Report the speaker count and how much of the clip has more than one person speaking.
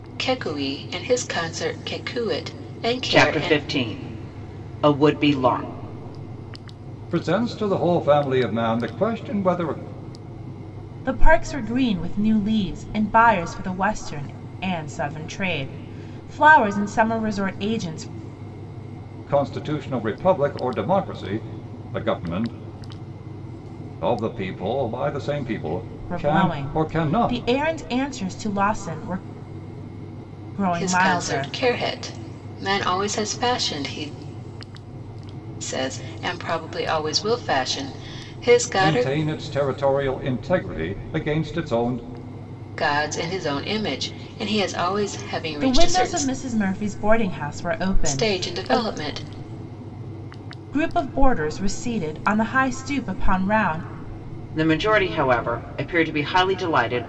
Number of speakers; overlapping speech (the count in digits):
4, about 8%